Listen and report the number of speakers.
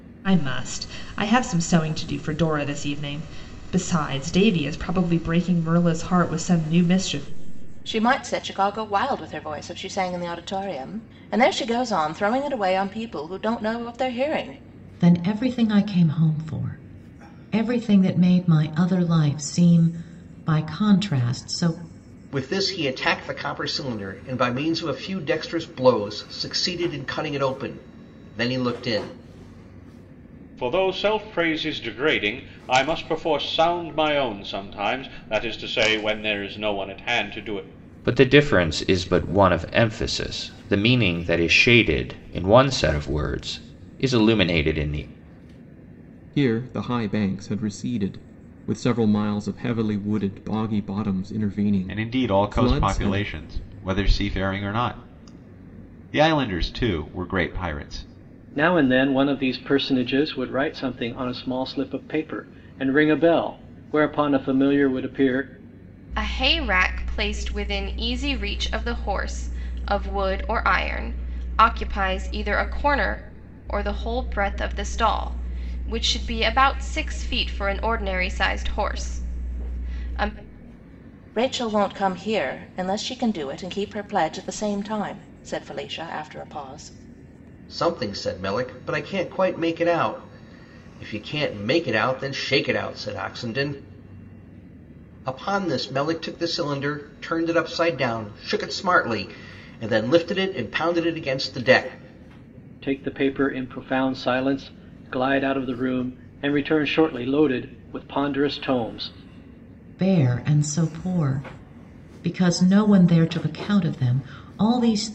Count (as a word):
ten